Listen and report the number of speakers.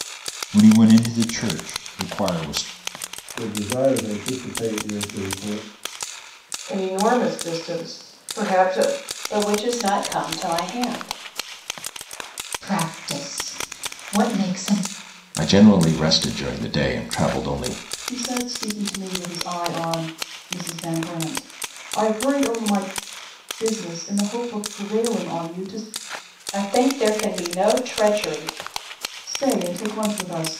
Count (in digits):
7